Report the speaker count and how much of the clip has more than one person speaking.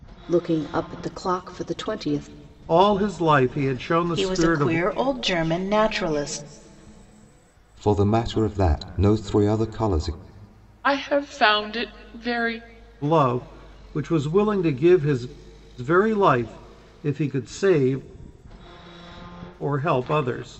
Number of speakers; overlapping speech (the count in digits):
5, about 4%